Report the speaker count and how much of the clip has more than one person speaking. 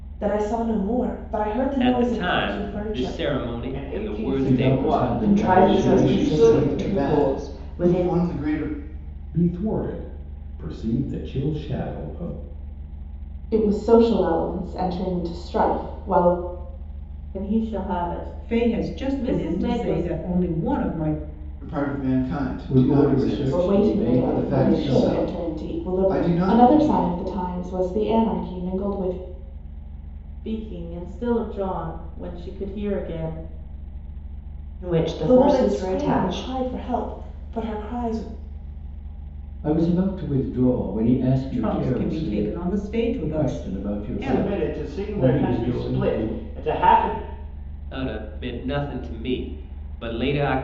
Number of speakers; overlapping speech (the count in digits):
10, about 35%